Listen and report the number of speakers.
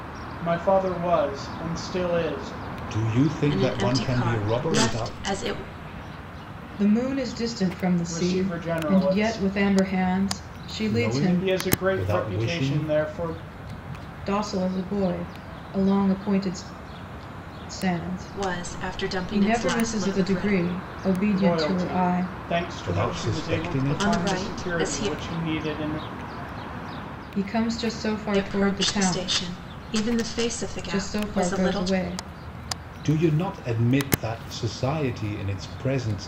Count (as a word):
four